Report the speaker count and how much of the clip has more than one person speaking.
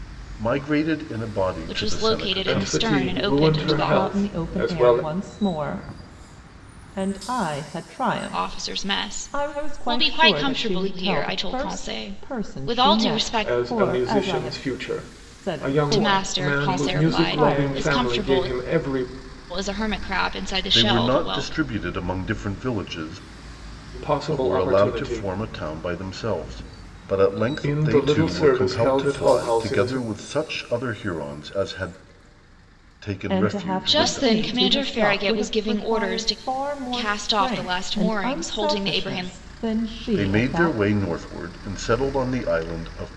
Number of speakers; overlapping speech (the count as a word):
four, about 55%